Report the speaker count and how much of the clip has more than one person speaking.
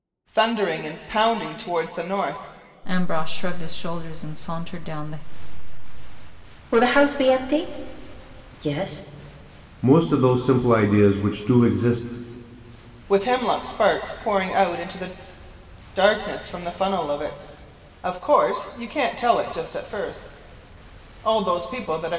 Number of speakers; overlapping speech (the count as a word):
four, no overlap